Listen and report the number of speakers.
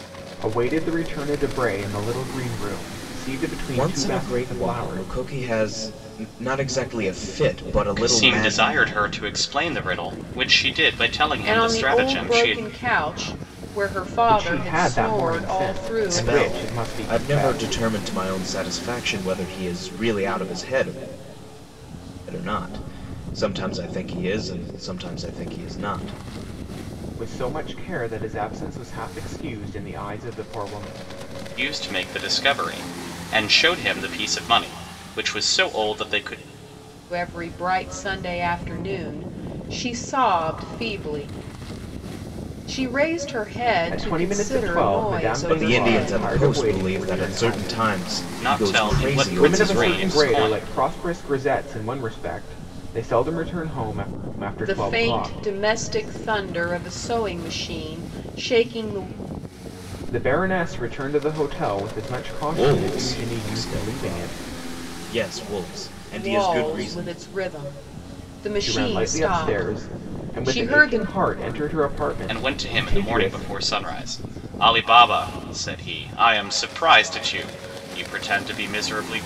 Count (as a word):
four